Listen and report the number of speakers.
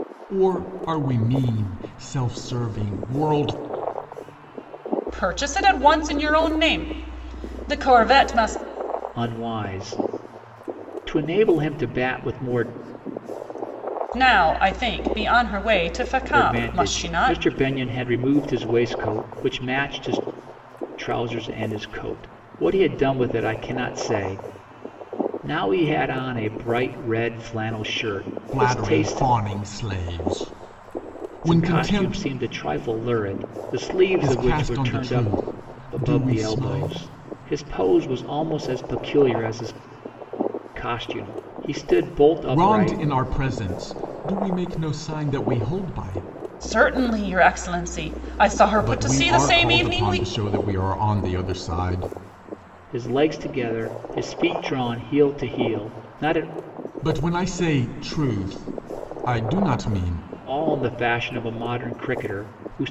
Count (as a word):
three